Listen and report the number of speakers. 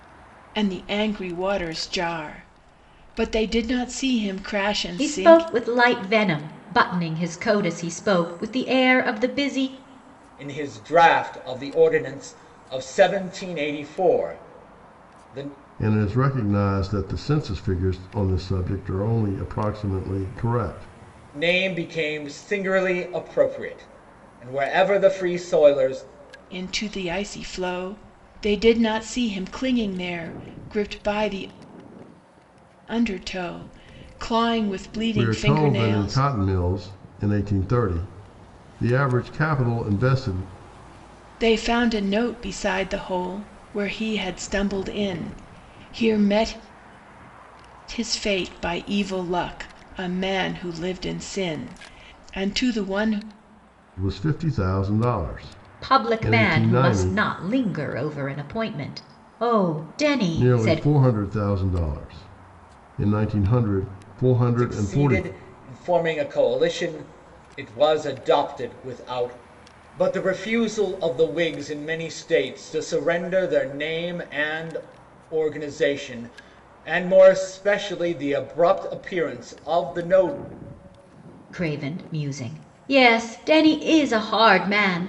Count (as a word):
four